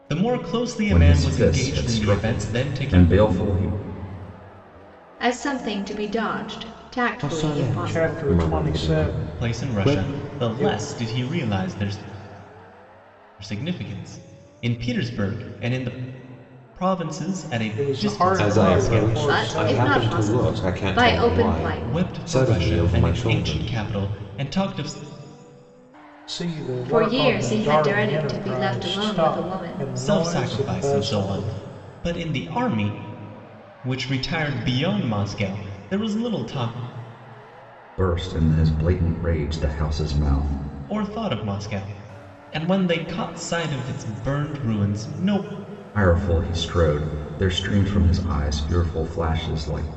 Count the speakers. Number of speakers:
five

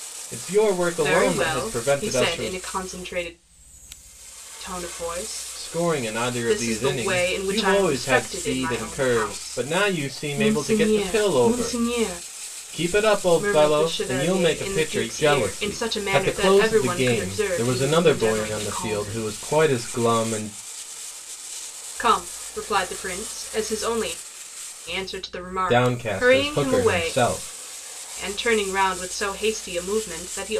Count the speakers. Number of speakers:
two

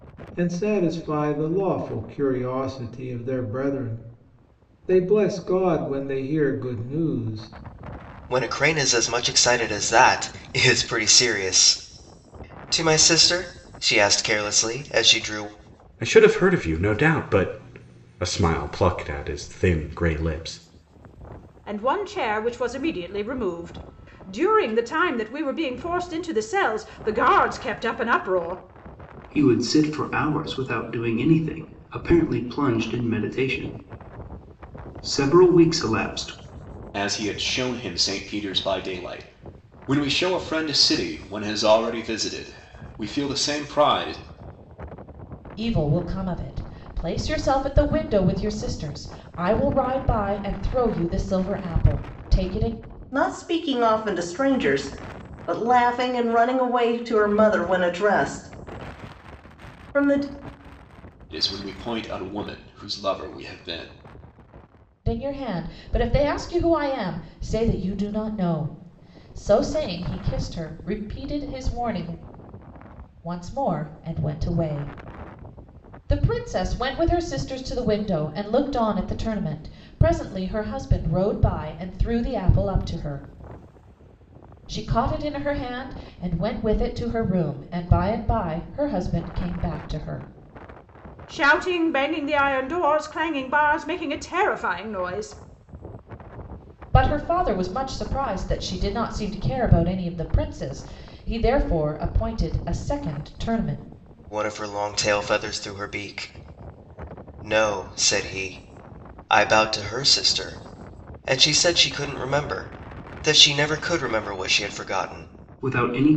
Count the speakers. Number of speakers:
eight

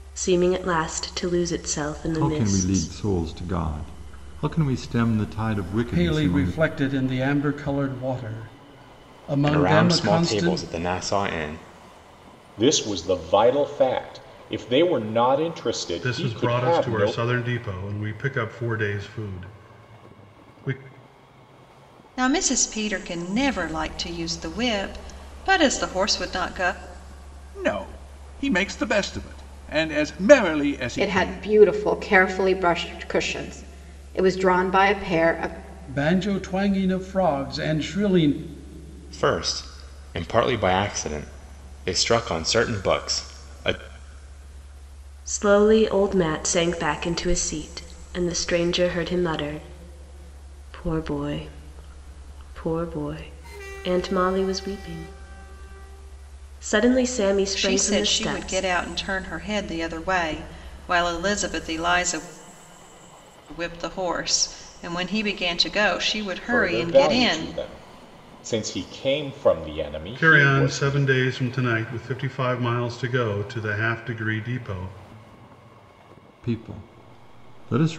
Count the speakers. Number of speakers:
nine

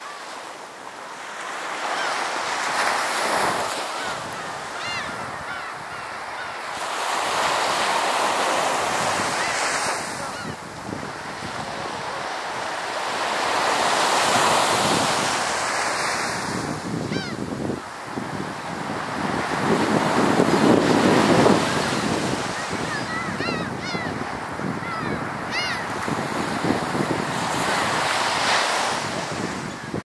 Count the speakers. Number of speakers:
zero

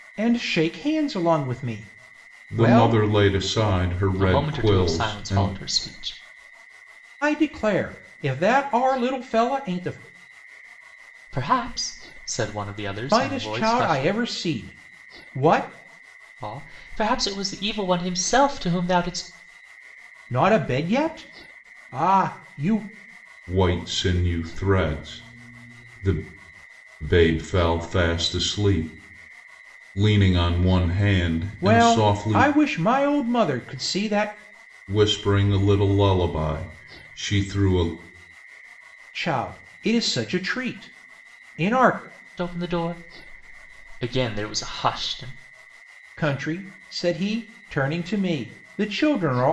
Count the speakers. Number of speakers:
three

